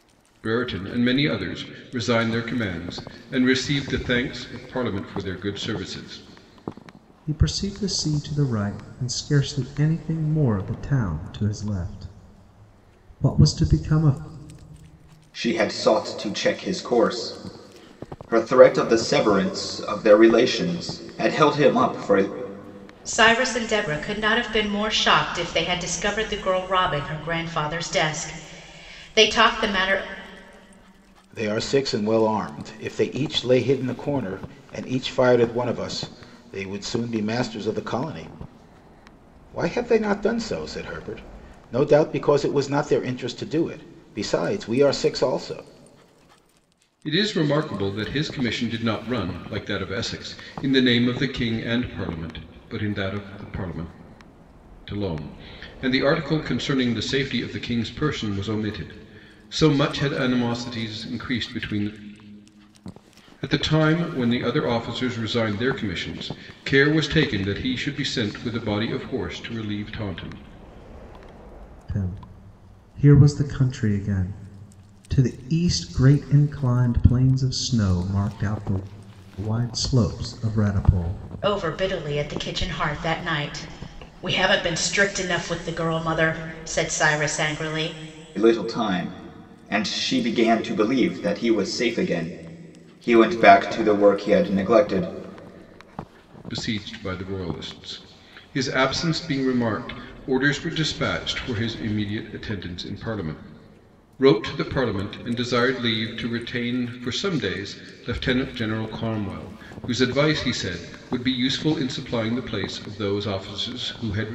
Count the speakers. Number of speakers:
five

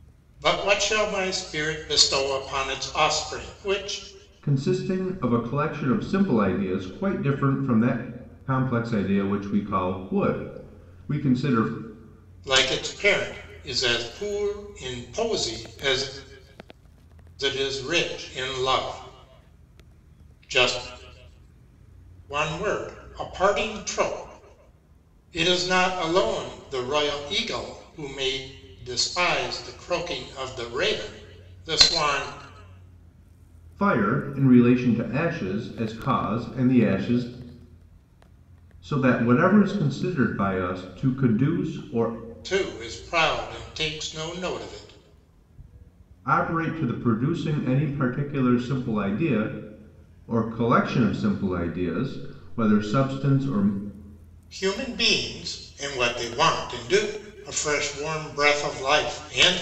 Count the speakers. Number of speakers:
two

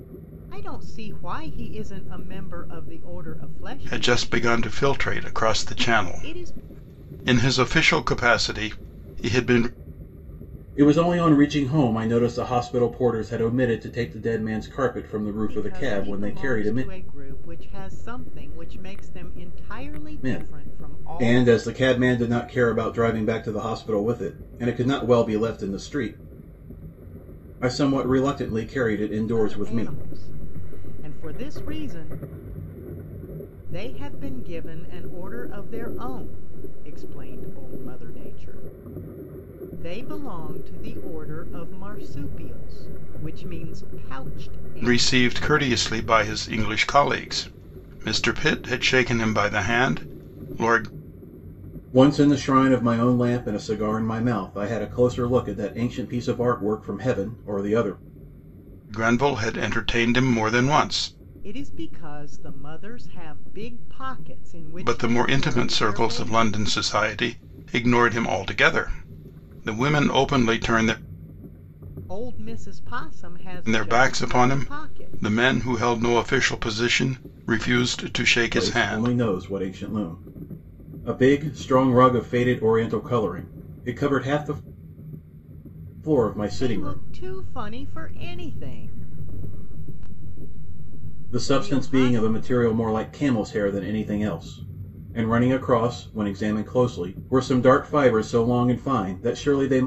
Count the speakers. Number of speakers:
three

